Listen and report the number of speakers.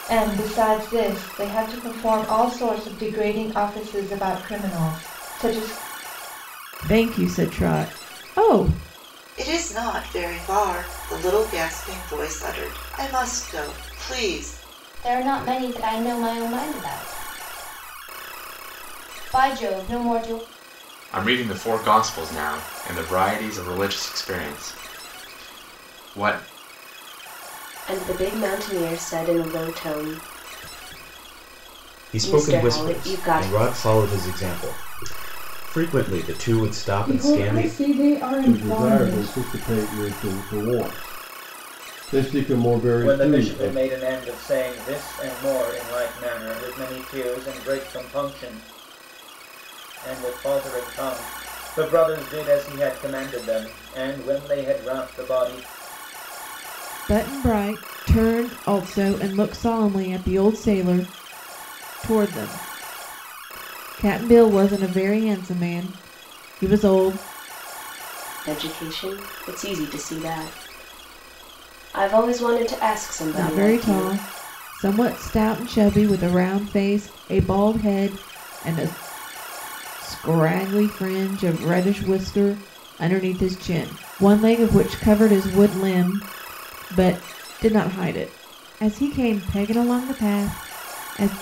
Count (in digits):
10